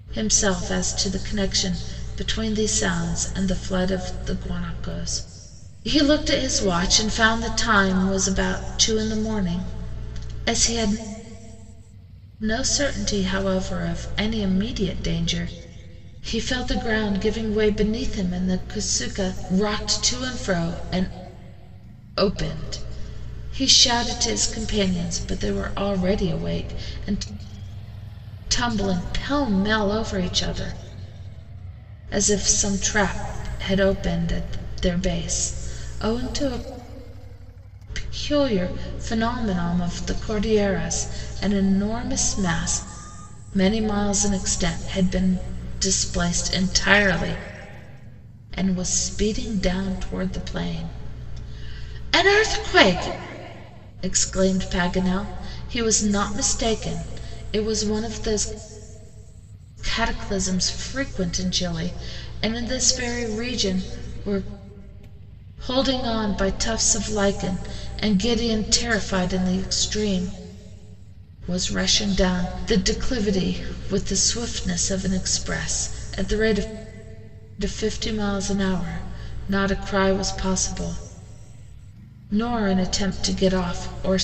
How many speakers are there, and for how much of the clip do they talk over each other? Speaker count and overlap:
one, no overlap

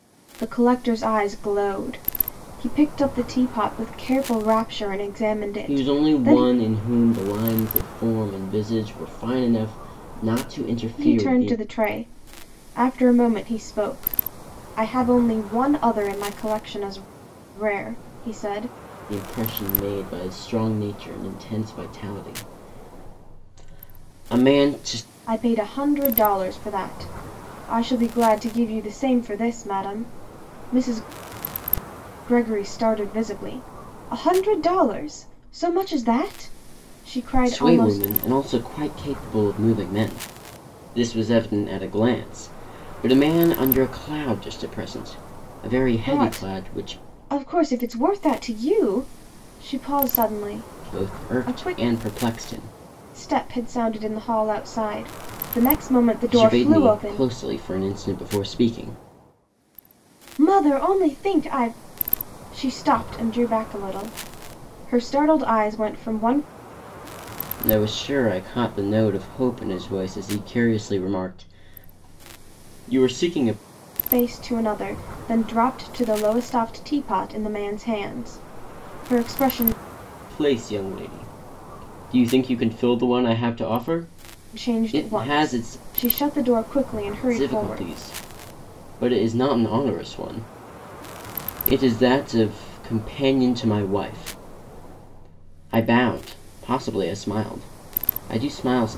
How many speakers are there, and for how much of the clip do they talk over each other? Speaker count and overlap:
two, about 7%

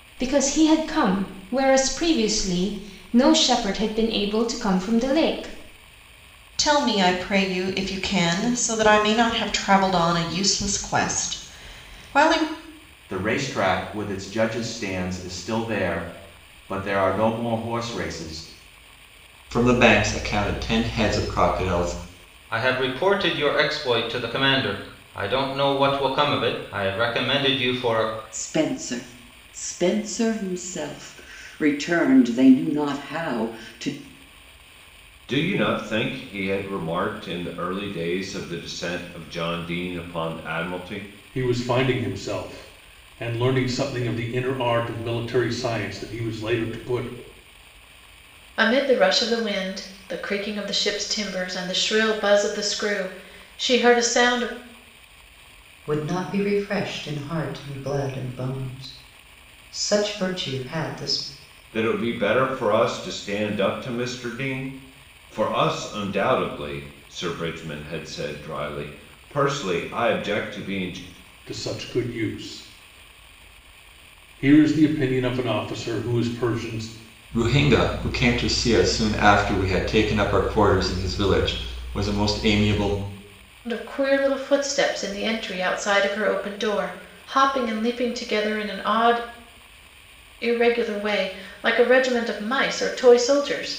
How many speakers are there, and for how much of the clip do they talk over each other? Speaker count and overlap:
ten, no overlap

